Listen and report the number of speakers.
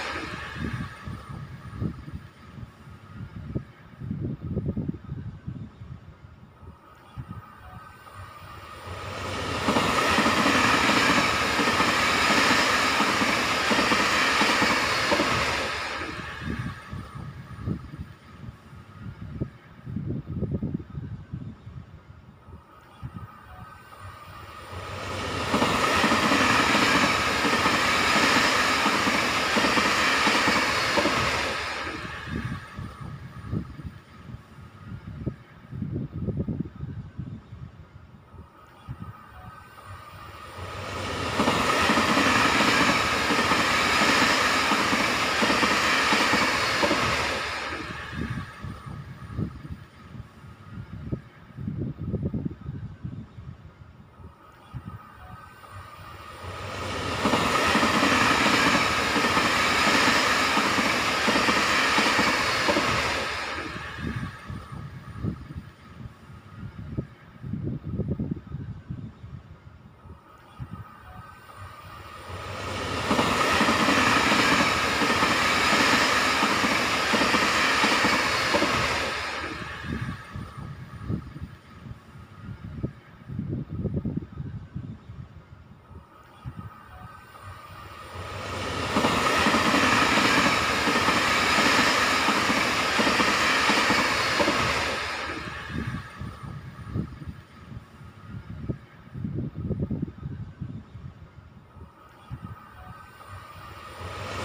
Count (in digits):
0